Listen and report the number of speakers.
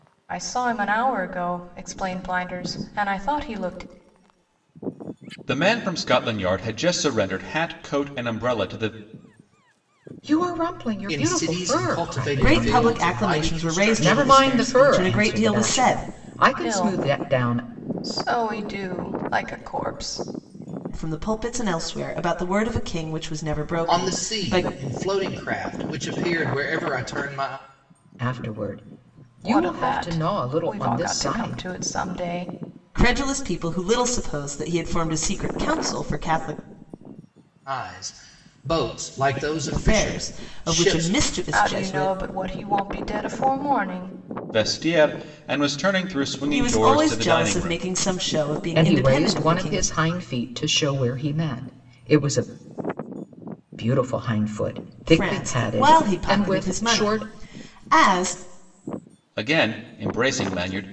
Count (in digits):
5